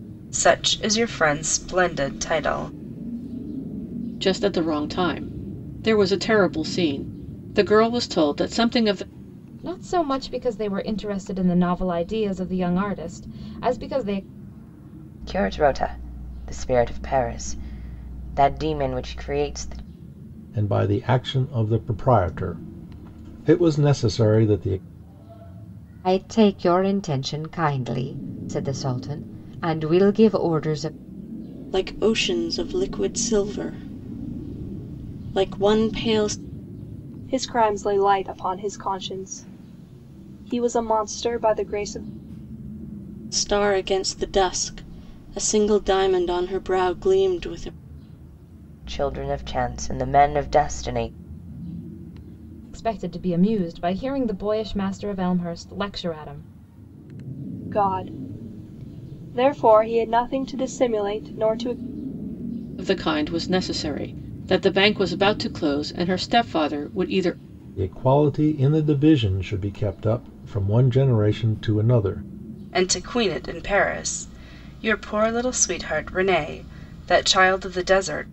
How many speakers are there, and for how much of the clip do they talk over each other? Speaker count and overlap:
eight, no overlap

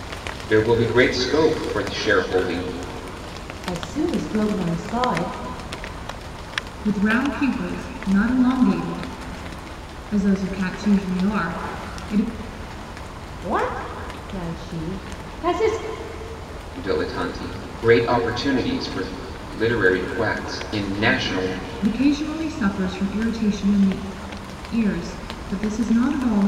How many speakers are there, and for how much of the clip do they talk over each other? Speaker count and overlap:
three, no overlap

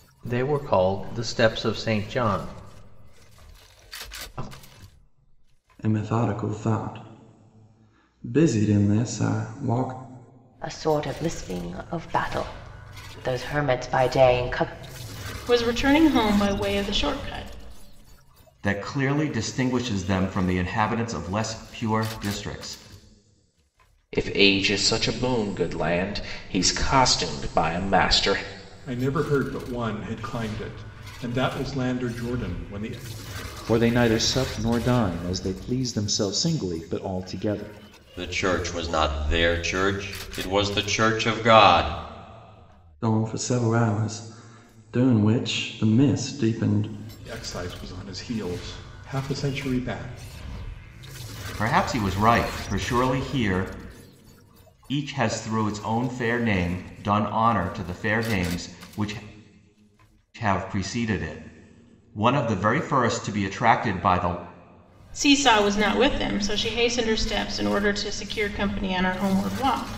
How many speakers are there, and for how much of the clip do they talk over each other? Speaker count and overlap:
nine, no overlap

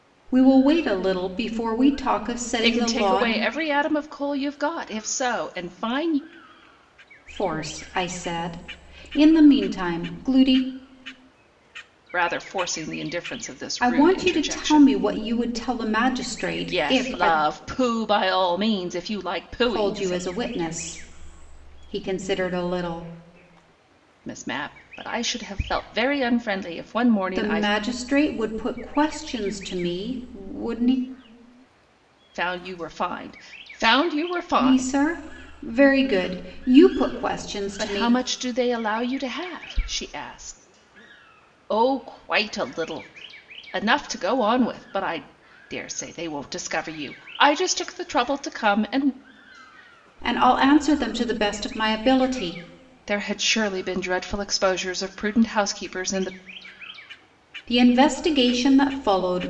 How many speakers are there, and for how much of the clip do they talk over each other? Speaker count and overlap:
two, about 8%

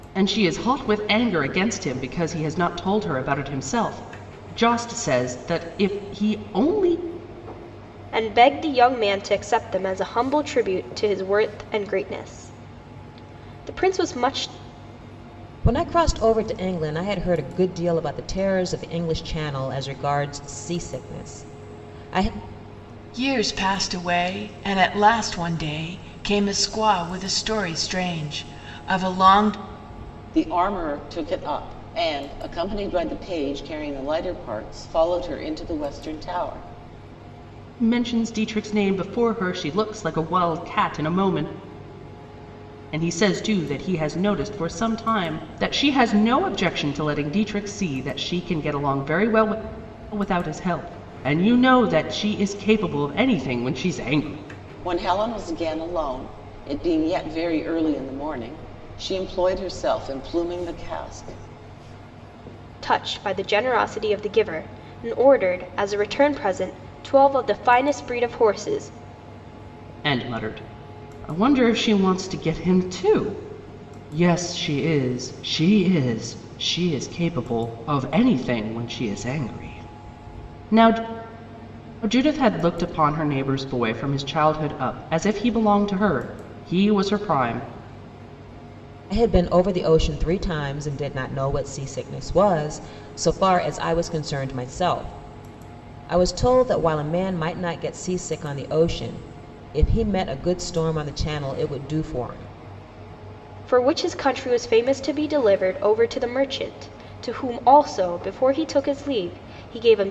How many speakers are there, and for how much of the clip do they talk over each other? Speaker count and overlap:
five, no overlap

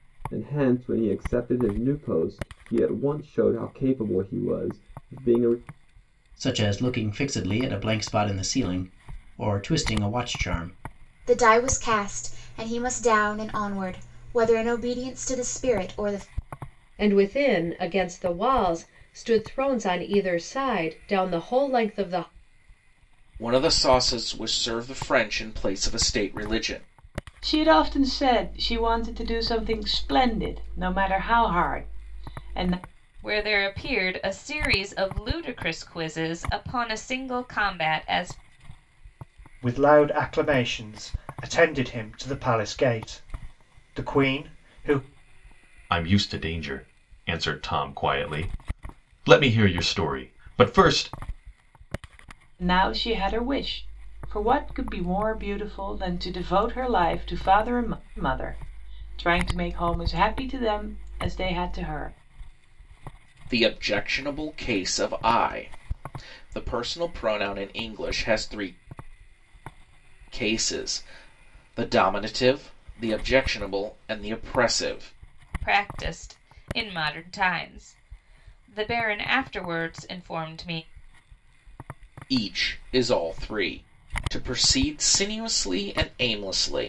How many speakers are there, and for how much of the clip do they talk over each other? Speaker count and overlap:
nine, no overlap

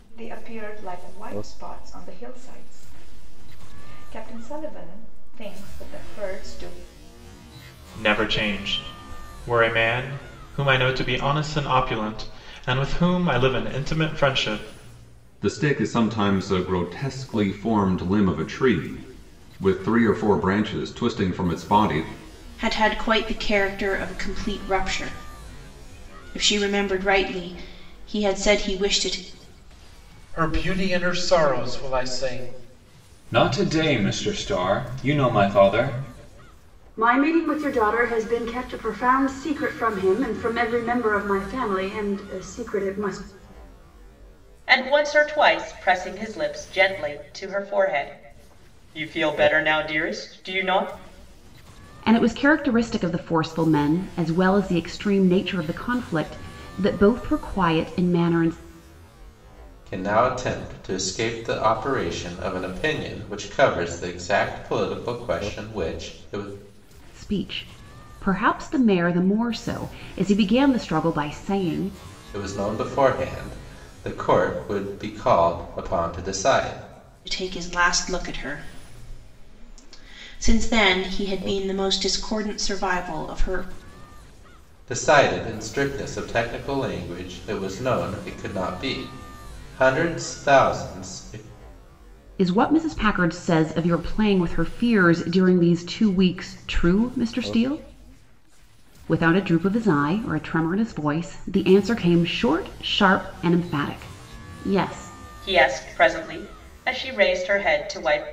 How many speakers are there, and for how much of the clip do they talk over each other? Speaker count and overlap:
ten, no overlap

